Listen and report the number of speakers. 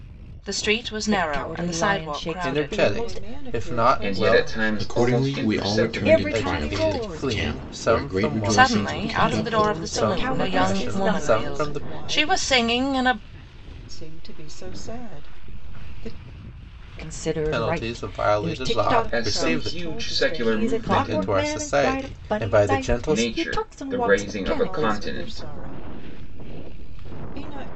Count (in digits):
6